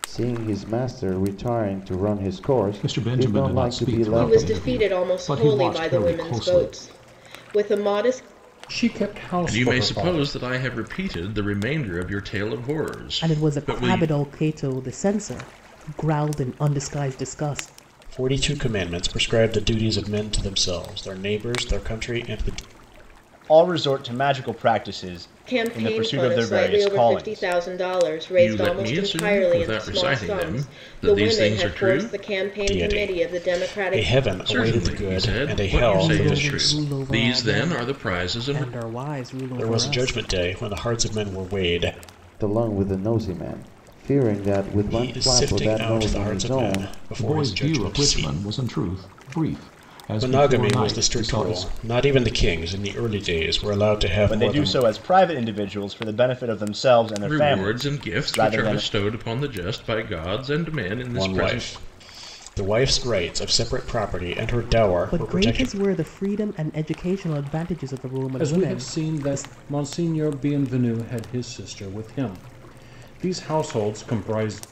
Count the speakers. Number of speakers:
8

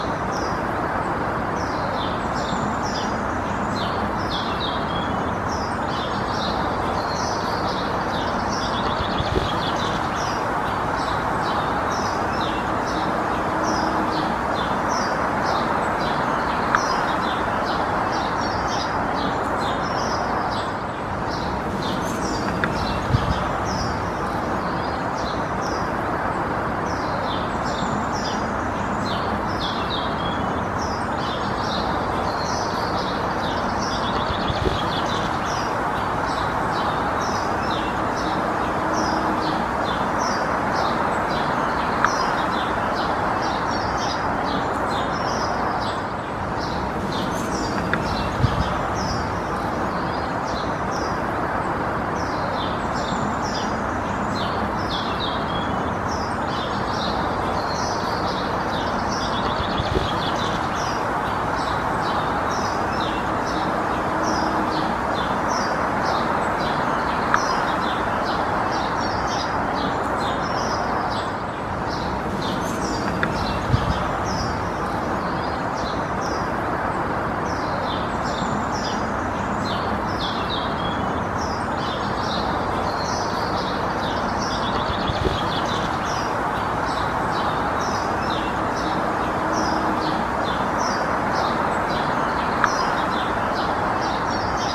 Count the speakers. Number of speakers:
0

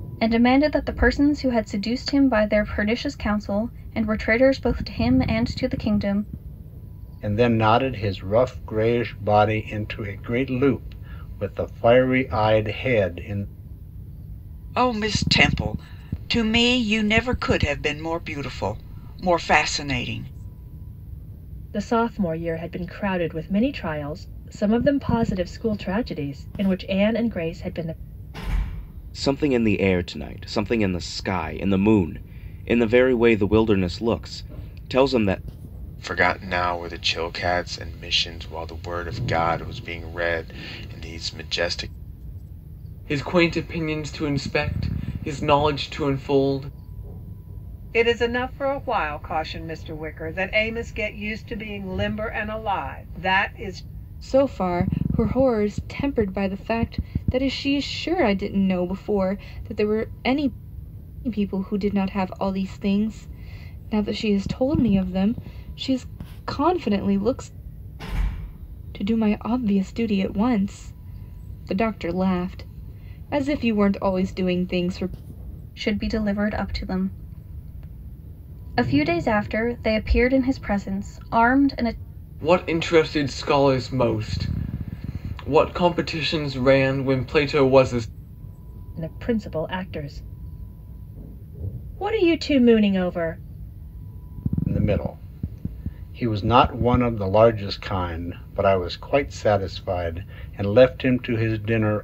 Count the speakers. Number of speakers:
9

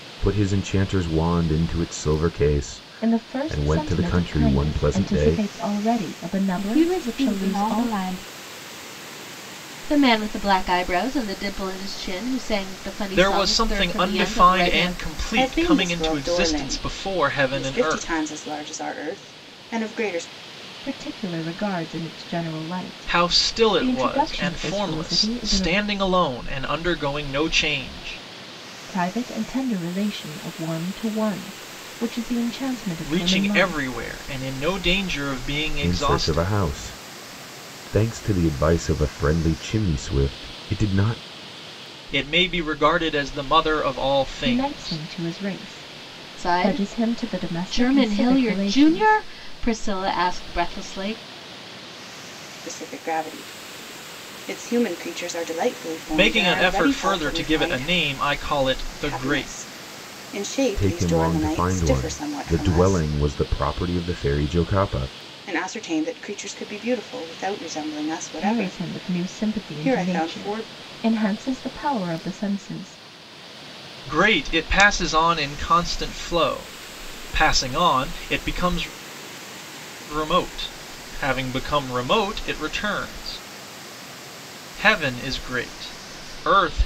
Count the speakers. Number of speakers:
6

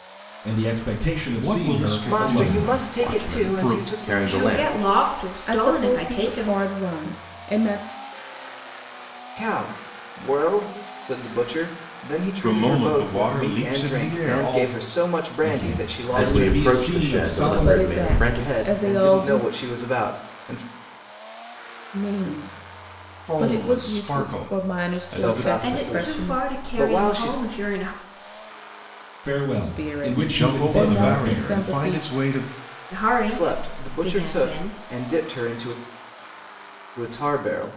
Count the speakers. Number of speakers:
6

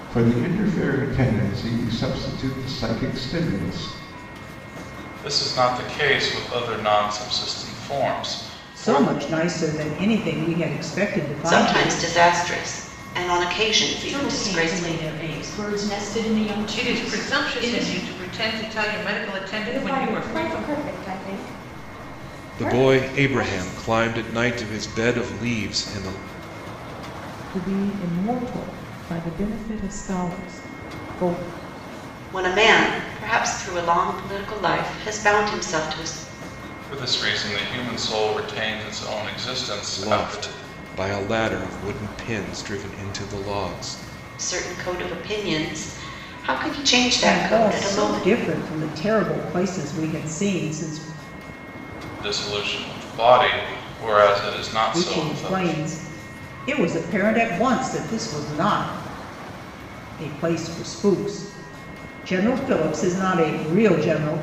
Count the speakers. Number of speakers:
9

